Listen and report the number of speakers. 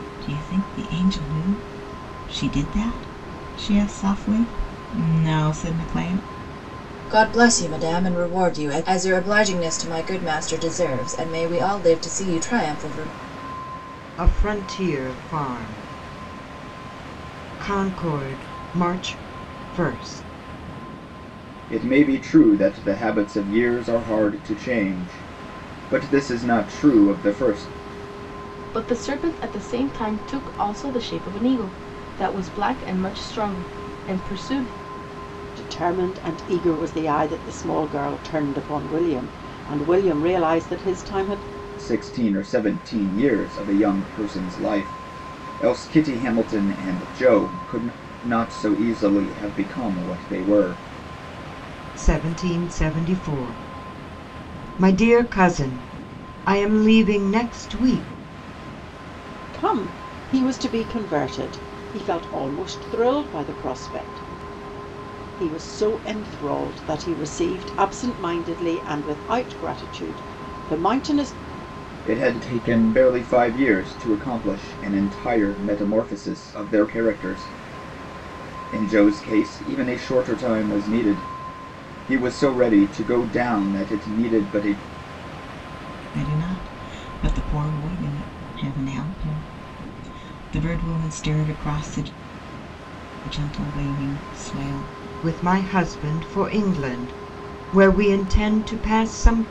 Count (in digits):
6